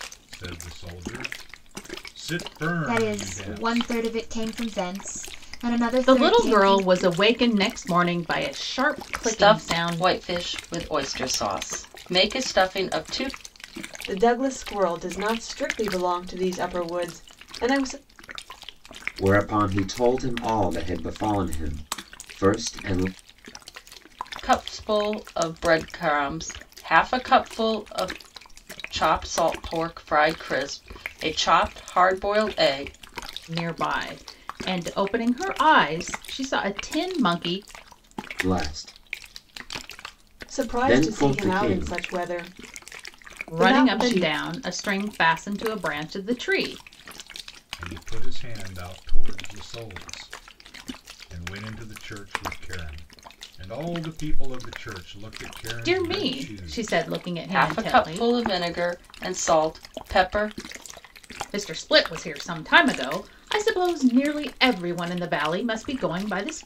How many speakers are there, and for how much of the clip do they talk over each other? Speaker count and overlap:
6, about 11%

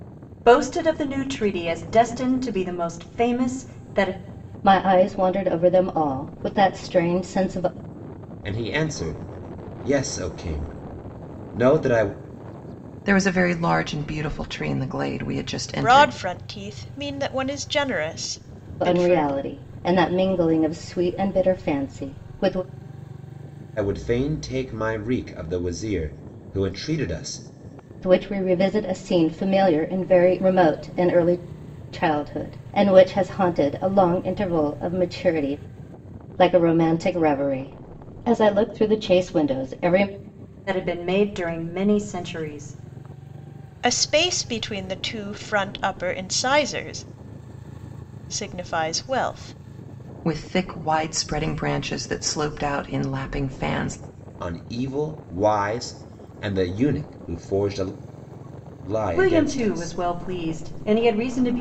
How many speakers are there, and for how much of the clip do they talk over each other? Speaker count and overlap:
5, about 3%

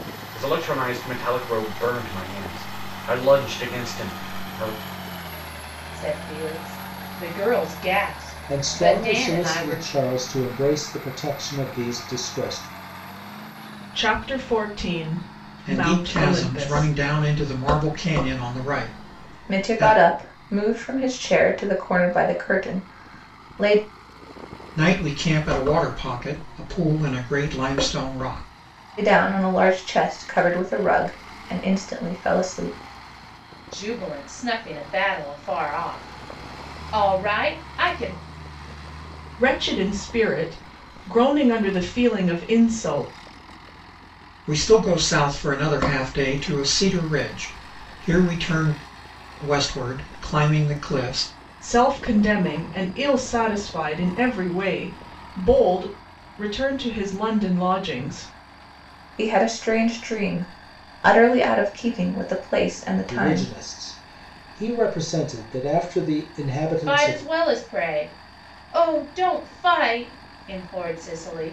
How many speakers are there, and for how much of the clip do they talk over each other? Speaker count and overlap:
6, about 6%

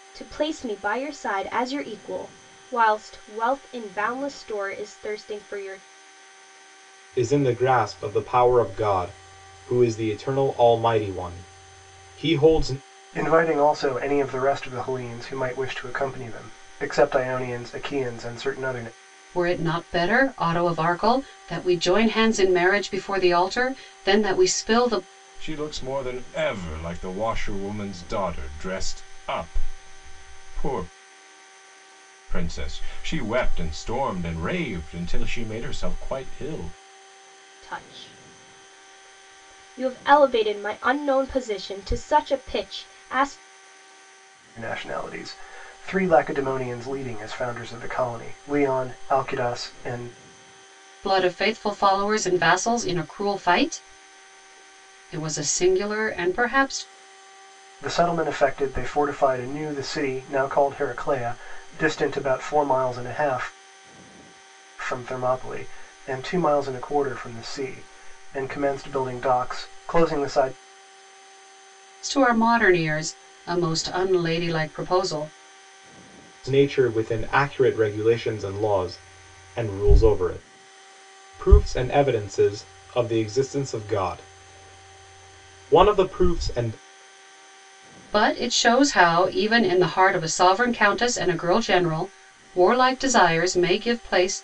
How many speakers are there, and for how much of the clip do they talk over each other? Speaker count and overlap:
5, no overlap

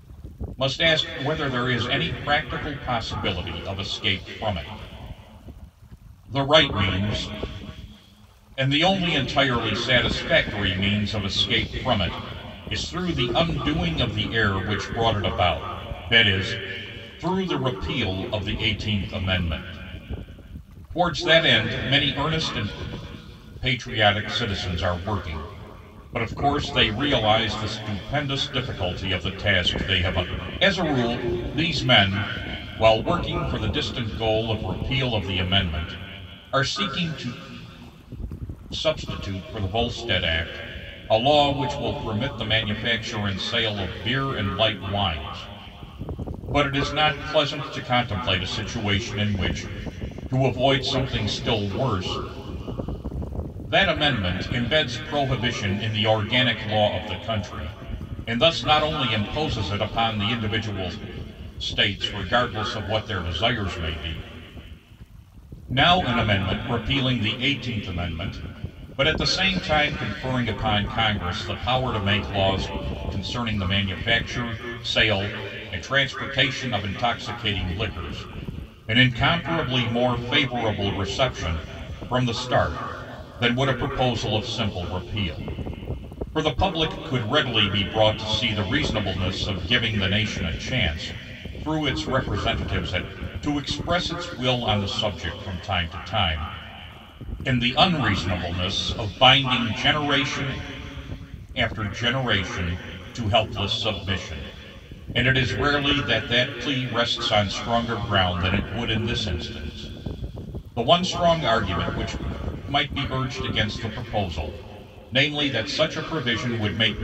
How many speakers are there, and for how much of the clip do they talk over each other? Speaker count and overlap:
1, no overlap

